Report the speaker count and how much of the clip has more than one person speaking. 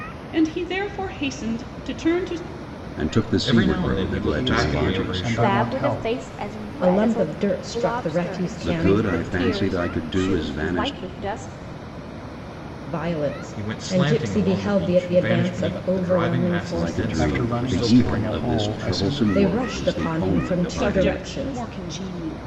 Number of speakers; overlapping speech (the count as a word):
six, about 64%